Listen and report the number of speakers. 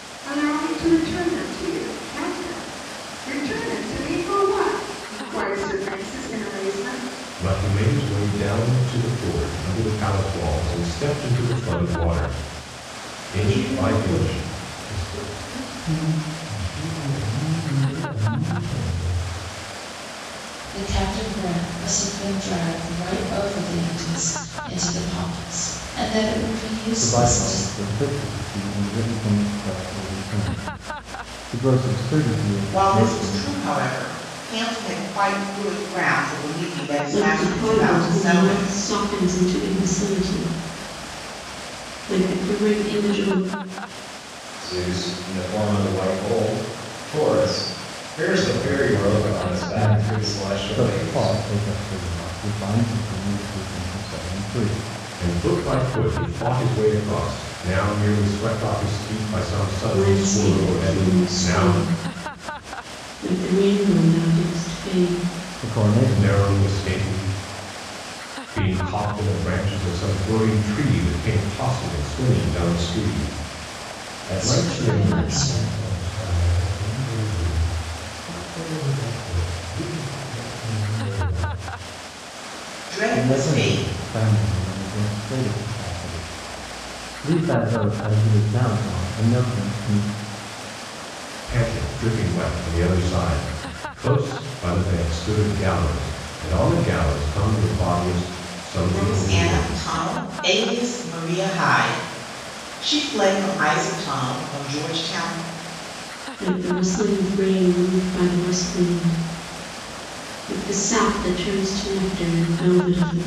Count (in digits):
8